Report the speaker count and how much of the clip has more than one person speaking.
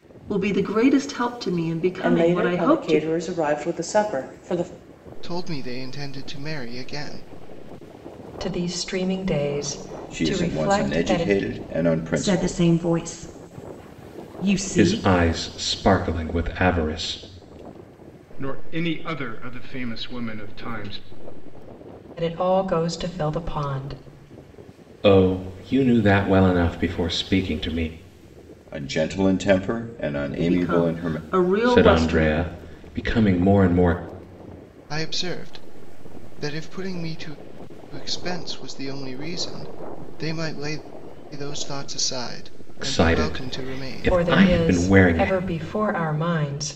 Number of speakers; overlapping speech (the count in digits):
8, about 16%